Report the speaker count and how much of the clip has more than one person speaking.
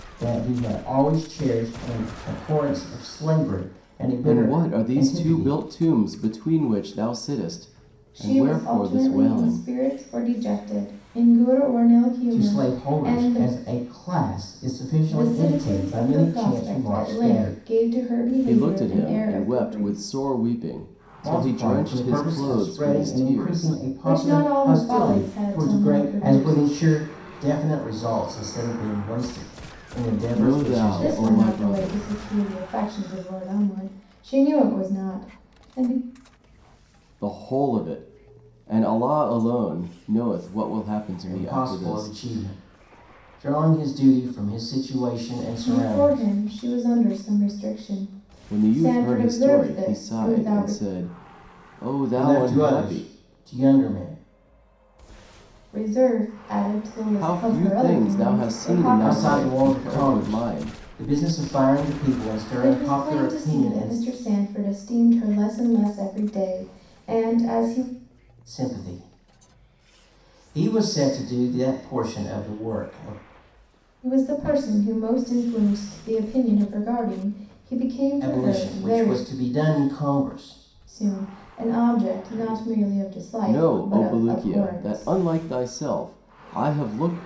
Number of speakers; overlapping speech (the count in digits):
3, about 32%